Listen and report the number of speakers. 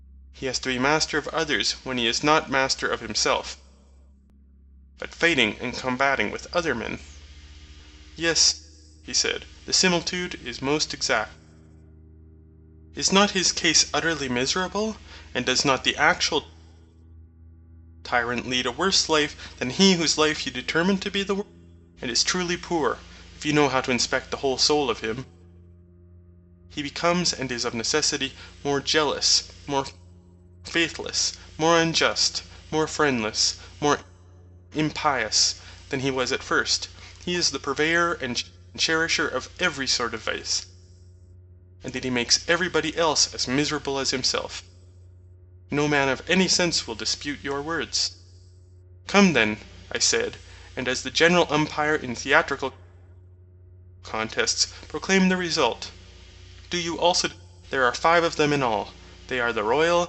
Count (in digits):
1